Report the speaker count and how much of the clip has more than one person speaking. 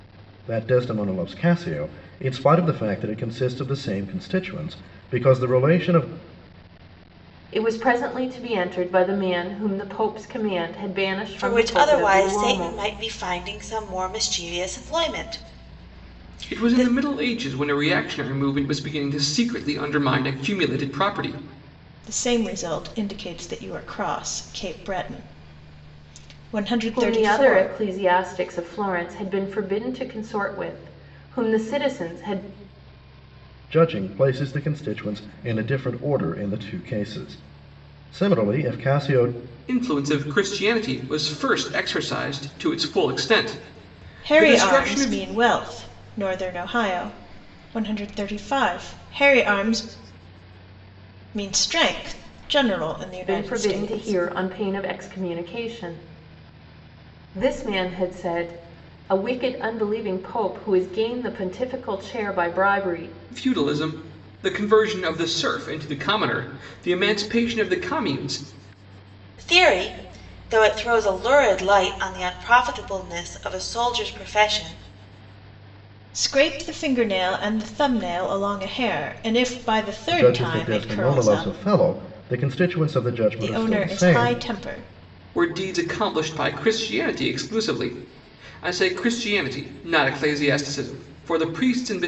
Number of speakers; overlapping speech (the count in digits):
5, about 8%